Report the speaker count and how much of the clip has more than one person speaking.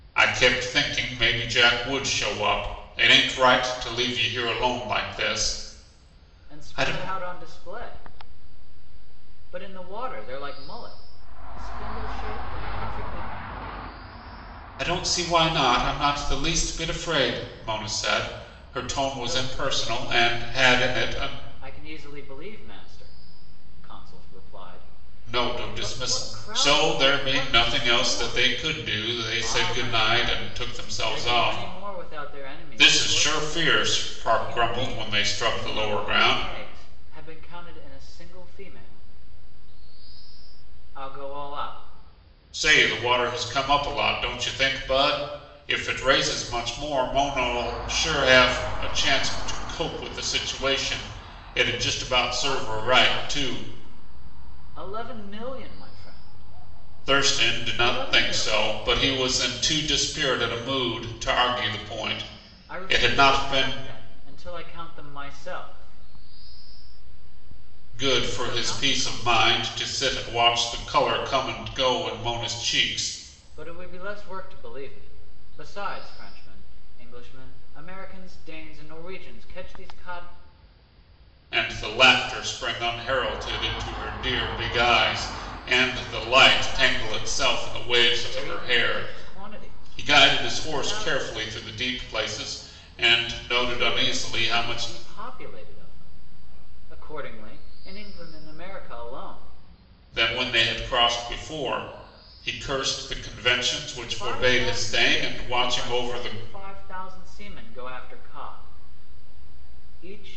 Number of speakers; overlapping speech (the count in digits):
2, about 25%